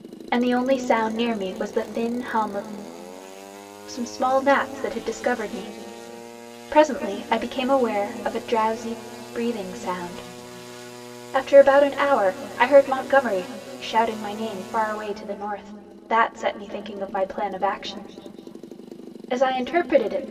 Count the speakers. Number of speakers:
1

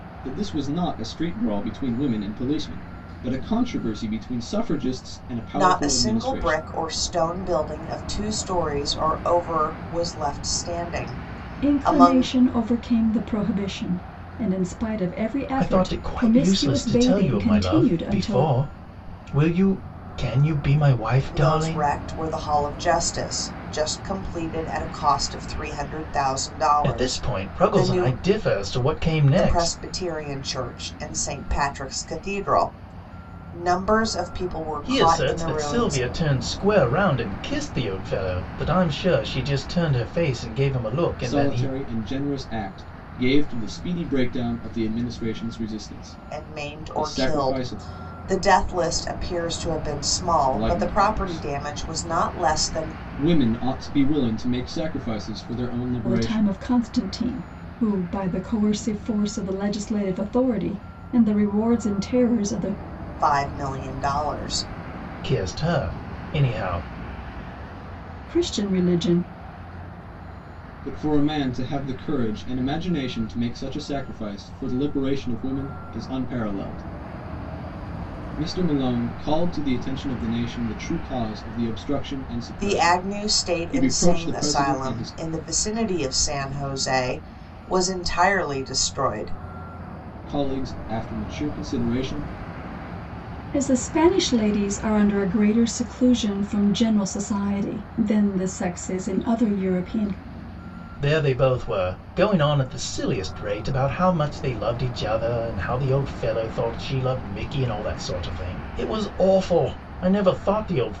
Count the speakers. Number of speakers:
4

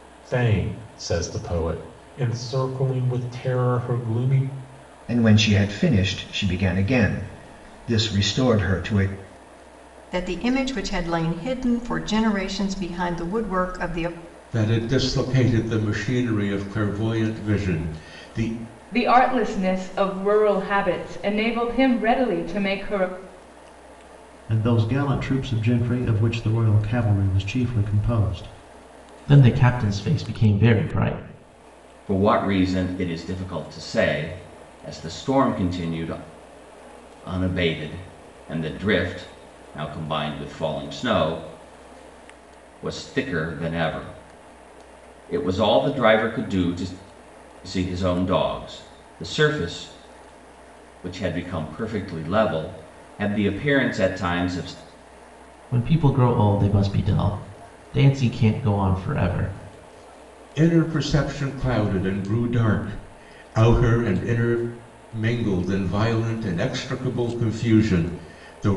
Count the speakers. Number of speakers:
8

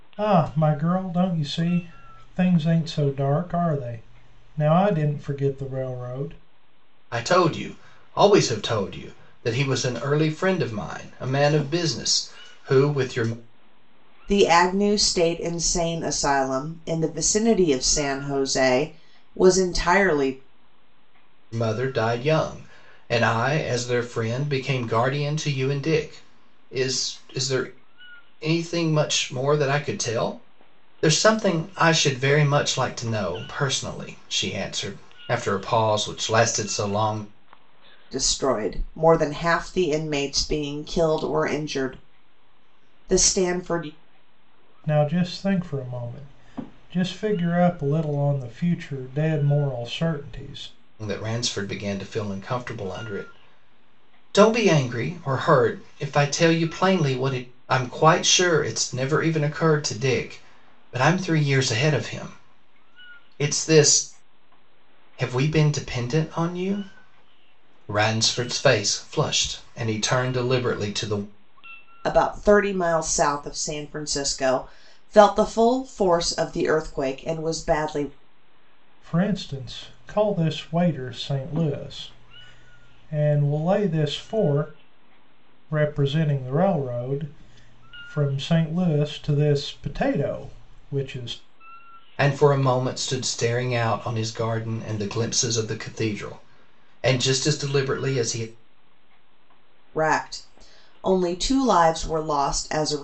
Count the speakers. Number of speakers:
3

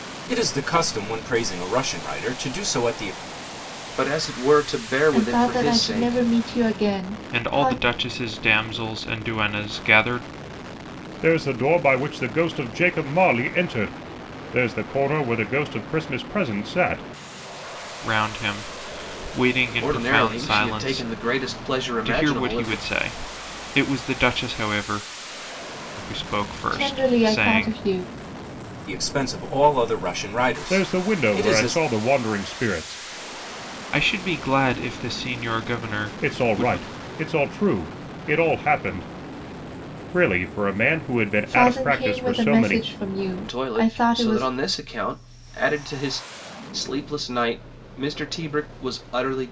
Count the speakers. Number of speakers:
5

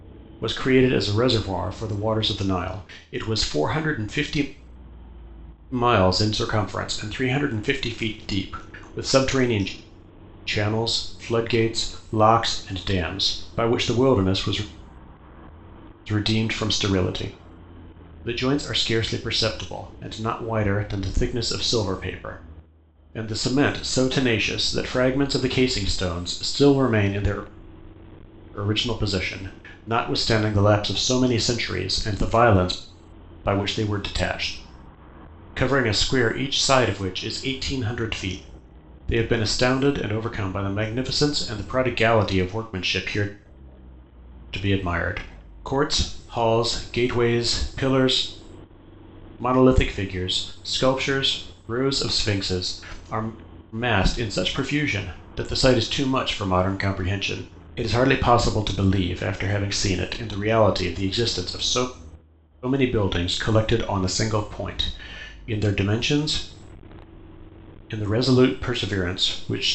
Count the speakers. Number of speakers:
1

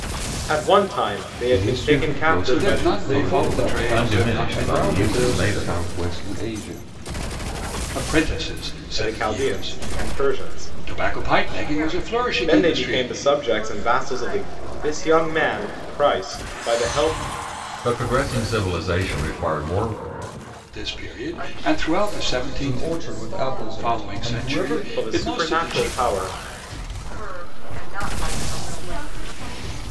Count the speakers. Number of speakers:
7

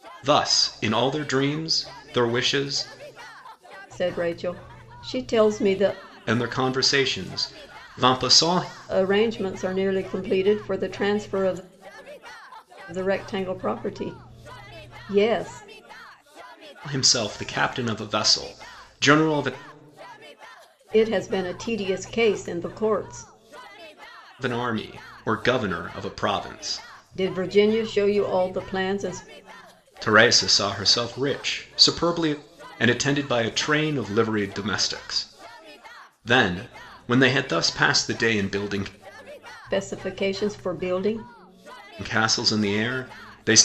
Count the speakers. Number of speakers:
2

